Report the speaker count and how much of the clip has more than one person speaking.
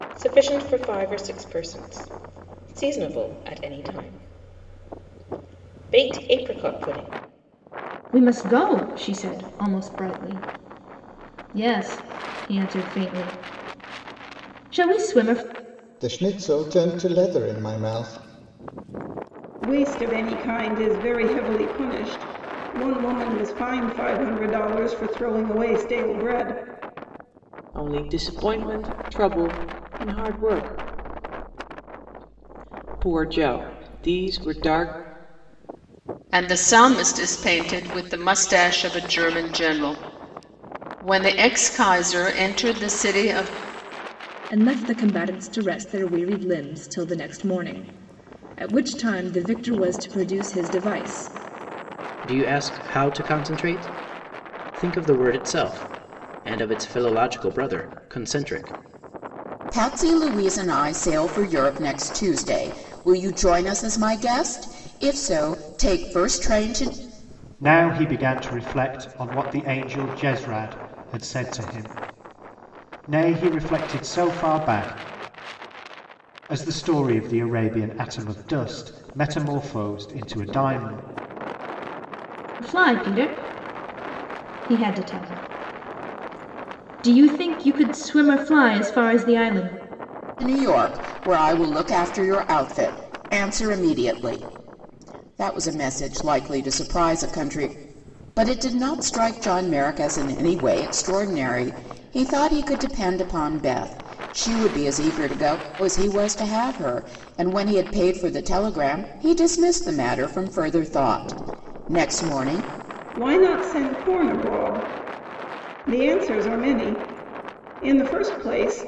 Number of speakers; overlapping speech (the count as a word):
ten, no overlap